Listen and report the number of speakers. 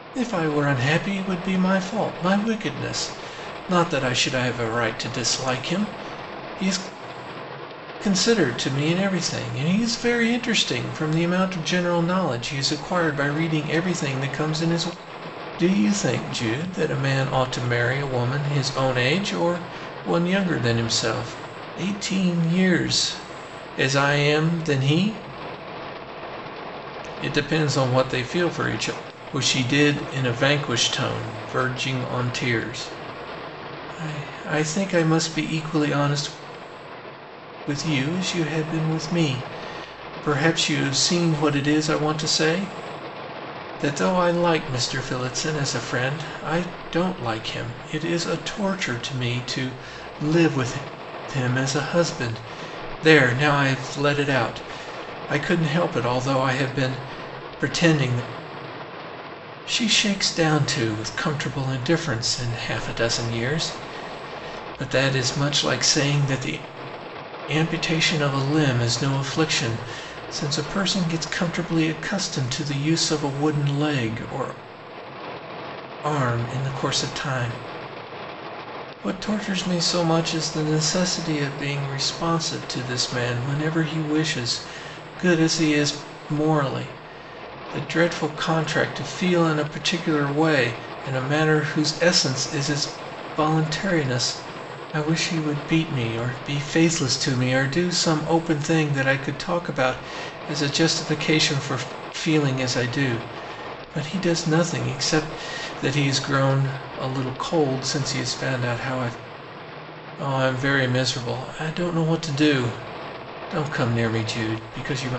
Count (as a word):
one